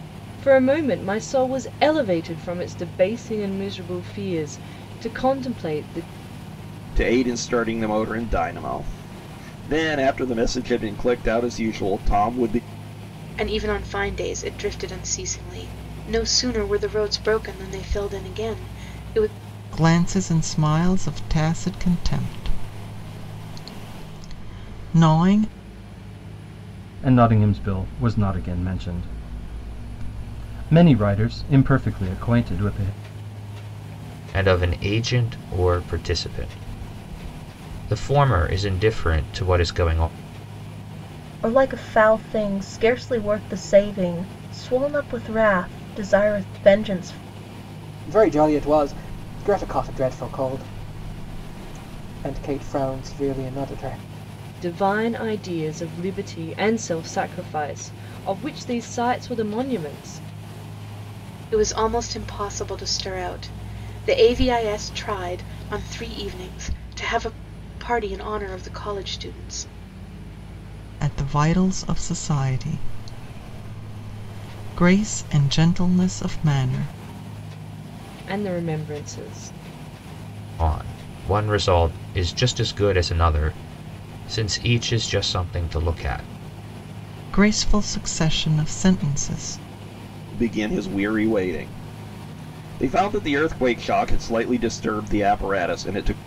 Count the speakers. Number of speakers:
eight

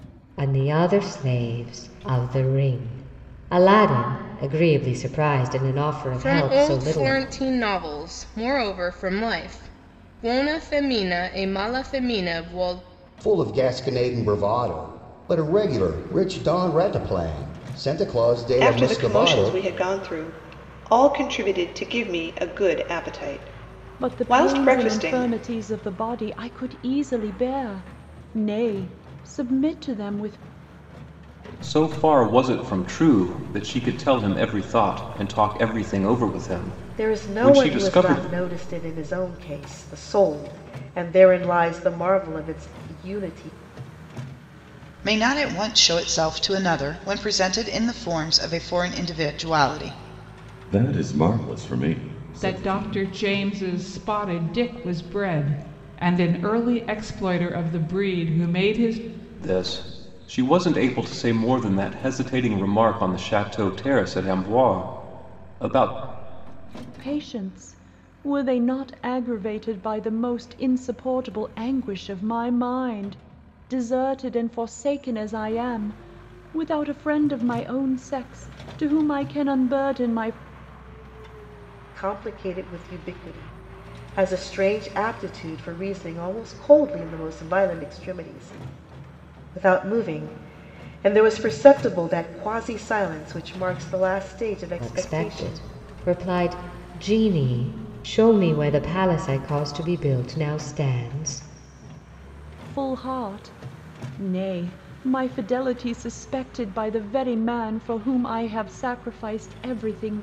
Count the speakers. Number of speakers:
ten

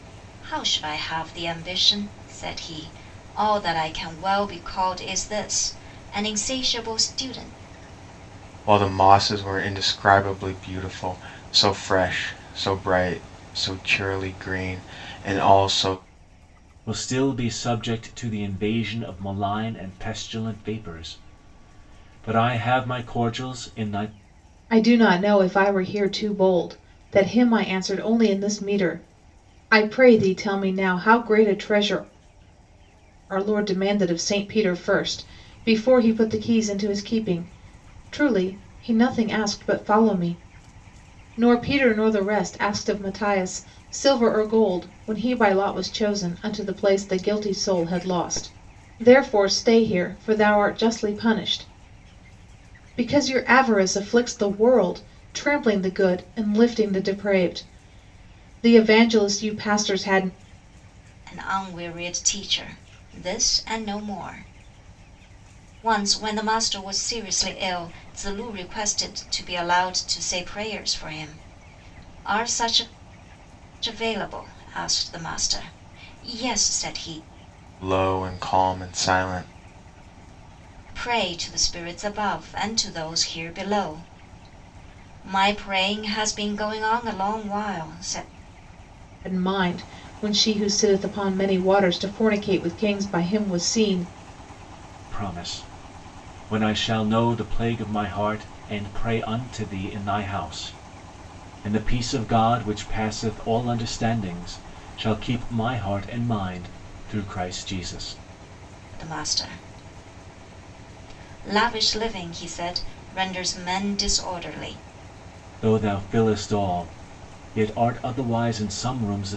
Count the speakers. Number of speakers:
four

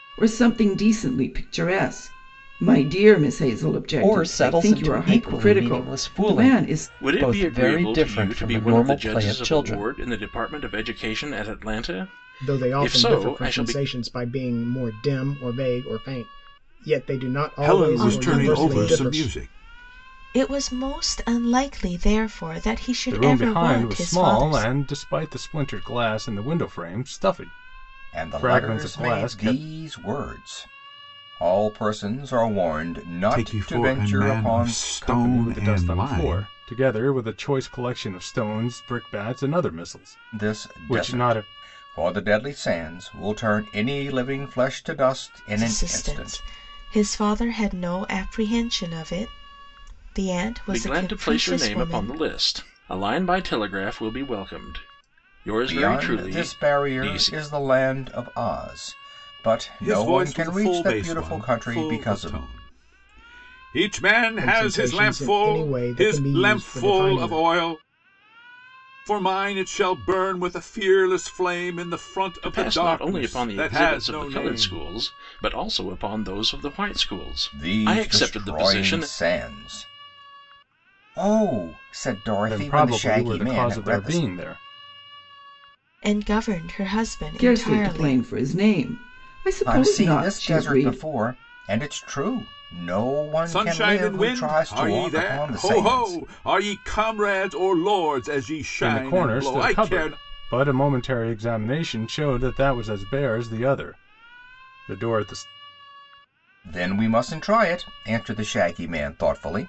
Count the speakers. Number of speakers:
eight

